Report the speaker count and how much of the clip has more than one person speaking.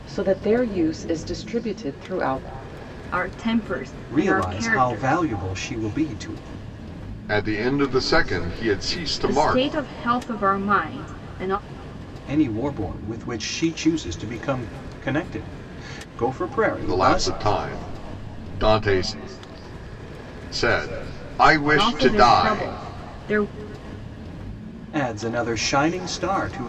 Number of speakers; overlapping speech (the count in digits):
4, about 12%